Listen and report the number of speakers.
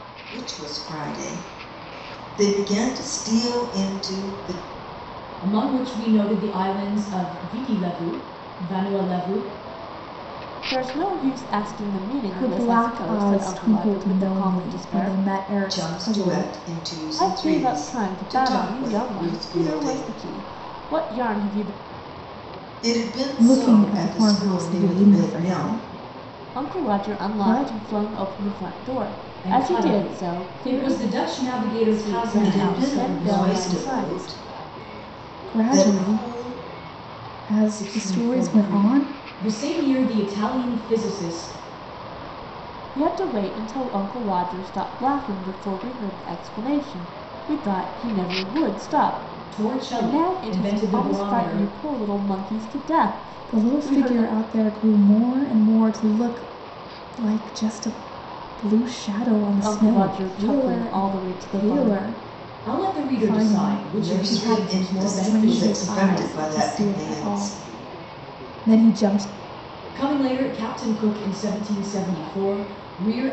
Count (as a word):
four